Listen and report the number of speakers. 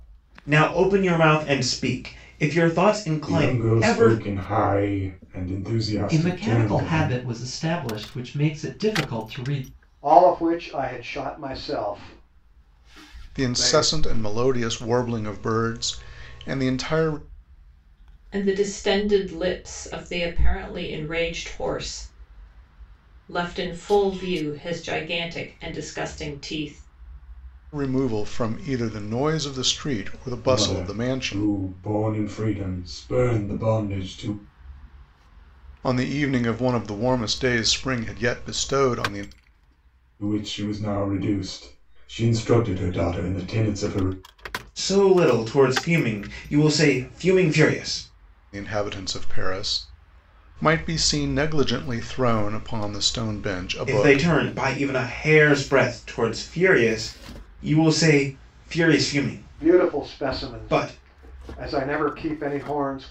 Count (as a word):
six